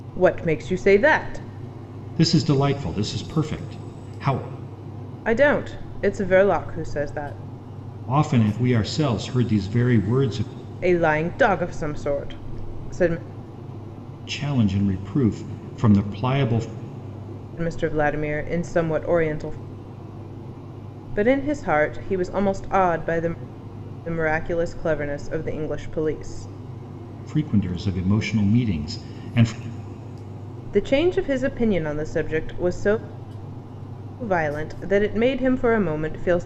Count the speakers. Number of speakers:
2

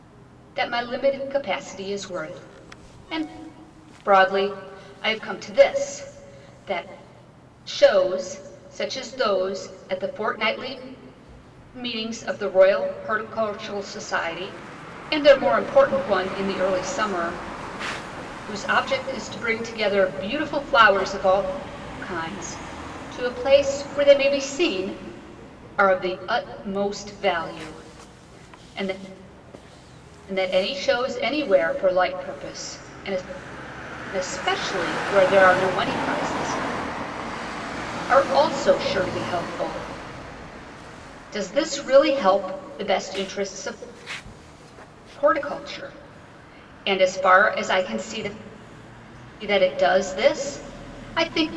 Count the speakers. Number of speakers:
1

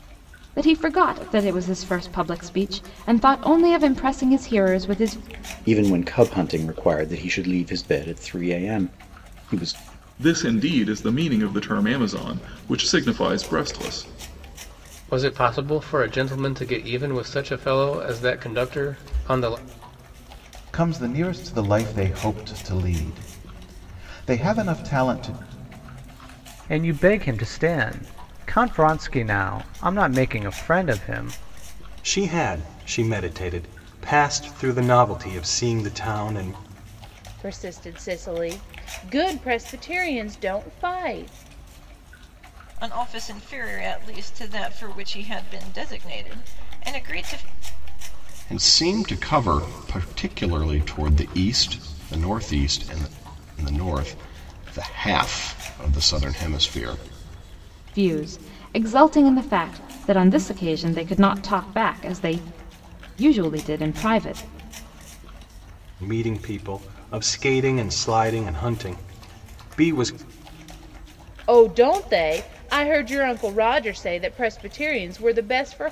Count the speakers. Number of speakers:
10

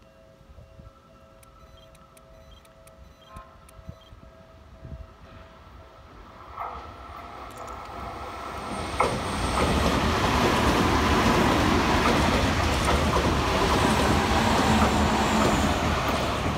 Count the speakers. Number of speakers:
0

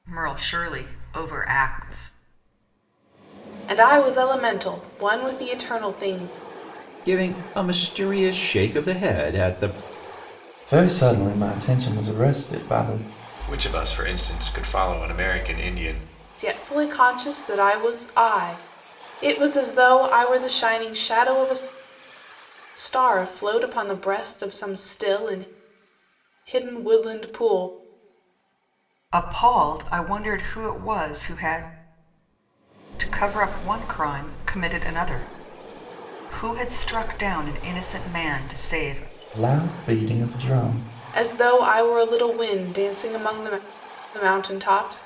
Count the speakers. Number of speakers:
5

